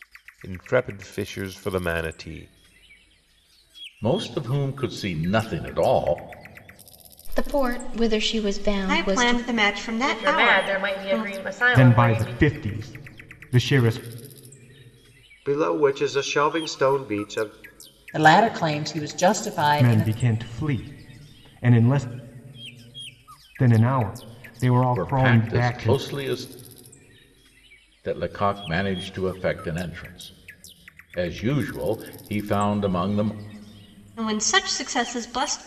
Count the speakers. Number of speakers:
8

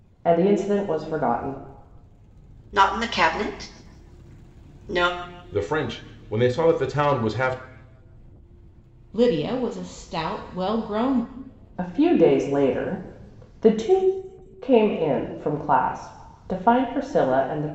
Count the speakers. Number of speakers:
4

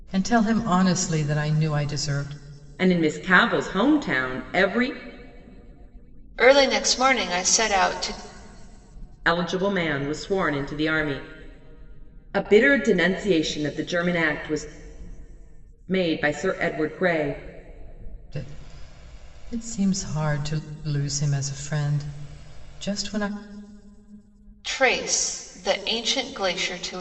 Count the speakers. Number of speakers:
3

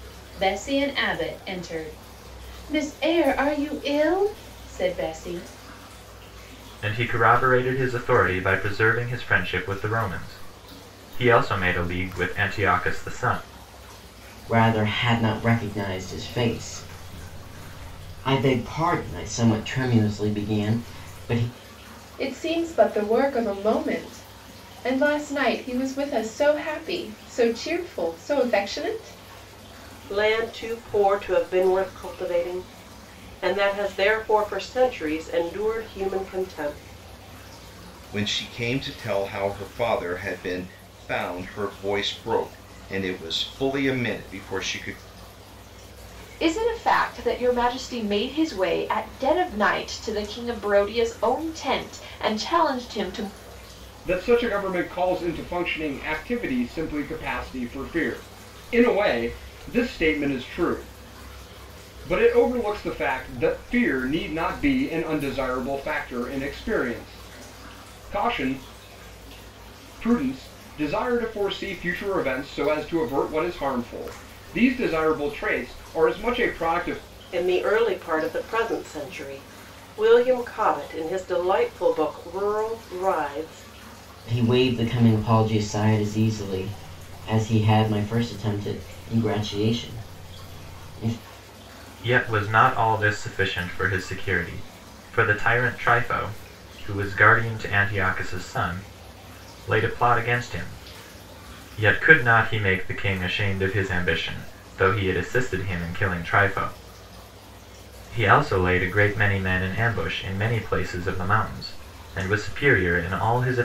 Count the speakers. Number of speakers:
8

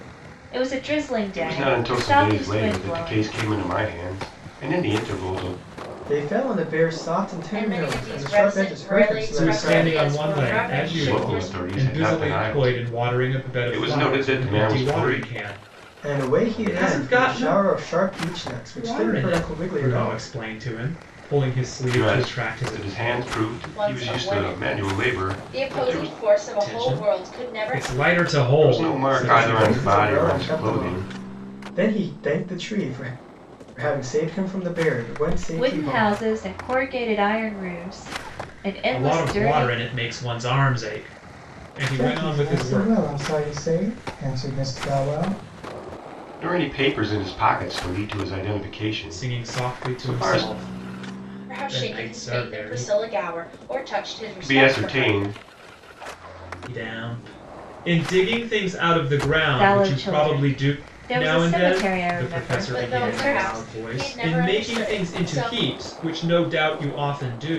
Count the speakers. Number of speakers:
5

